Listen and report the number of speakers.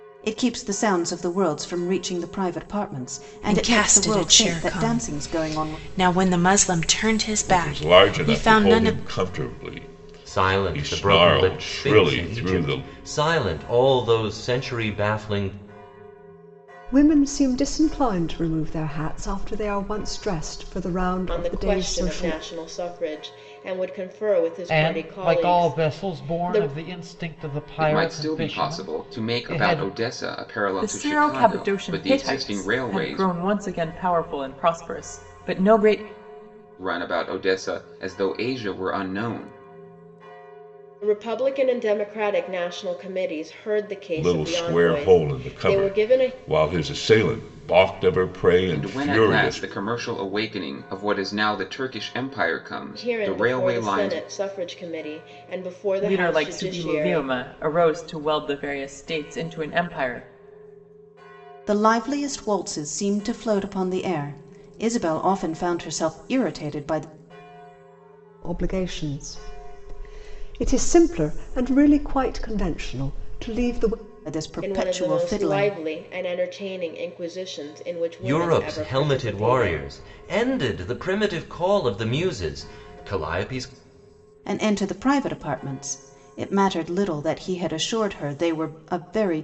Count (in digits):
9